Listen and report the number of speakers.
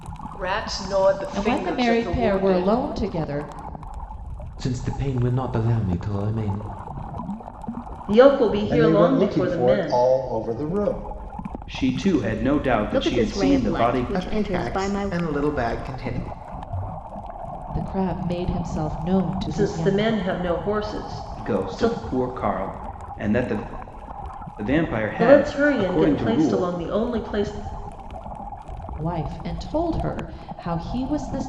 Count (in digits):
8